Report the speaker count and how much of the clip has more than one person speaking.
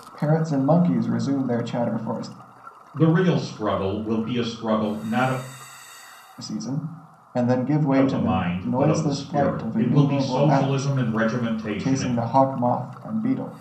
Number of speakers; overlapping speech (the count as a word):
two, about 23%